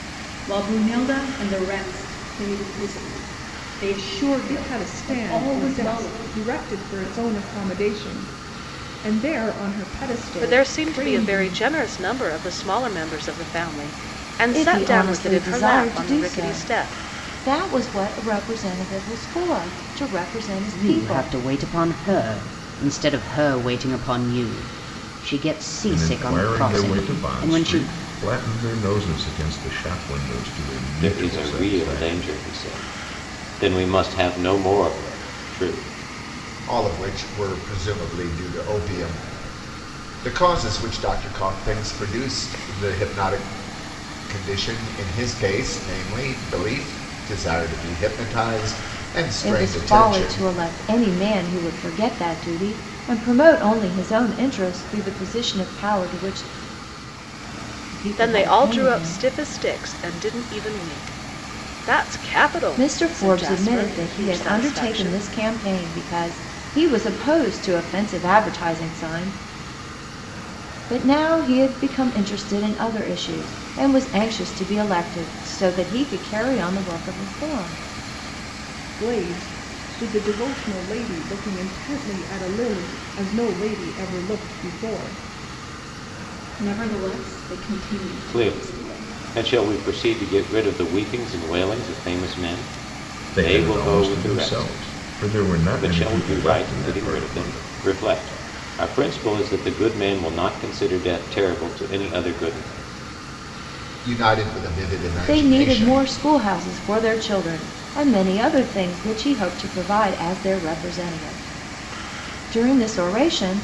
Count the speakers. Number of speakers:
eight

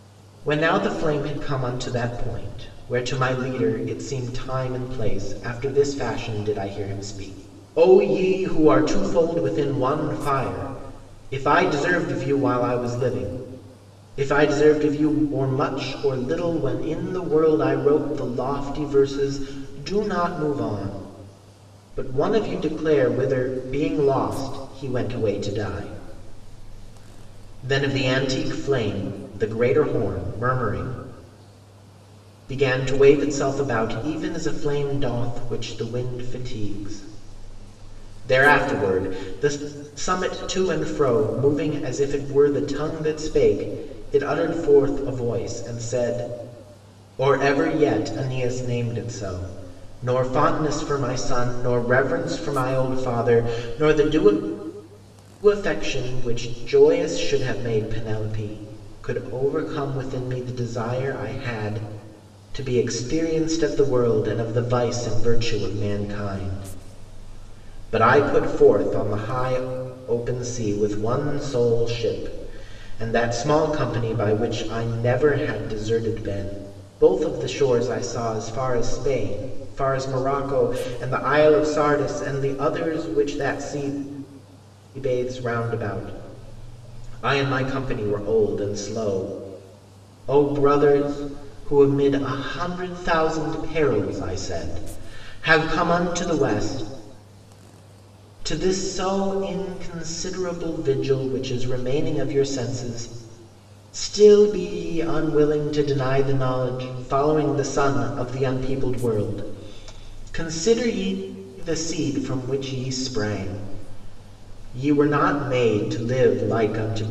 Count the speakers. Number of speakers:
one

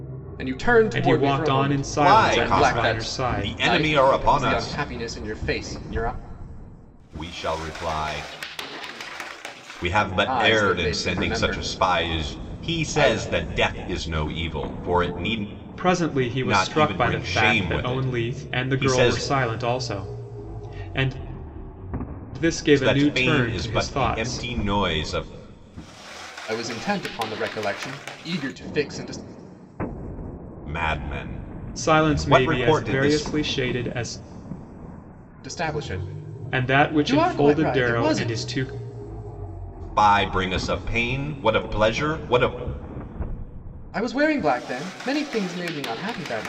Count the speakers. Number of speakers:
three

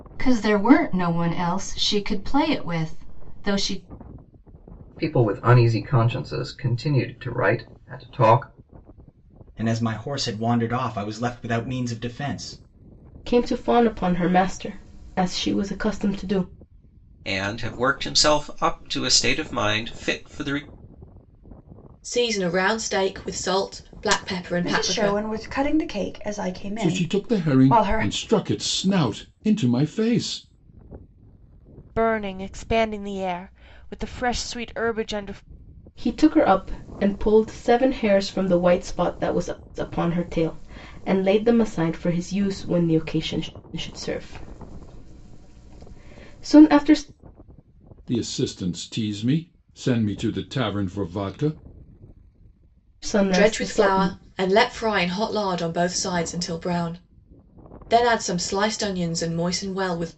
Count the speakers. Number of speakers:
nine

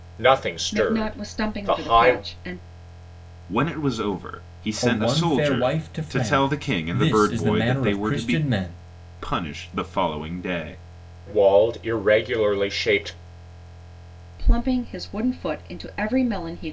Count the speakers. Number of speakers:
four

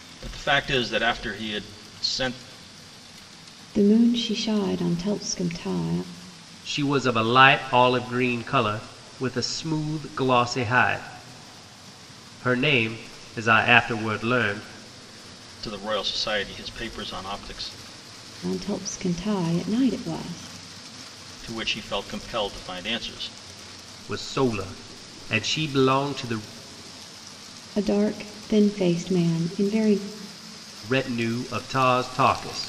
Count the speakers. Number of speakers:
three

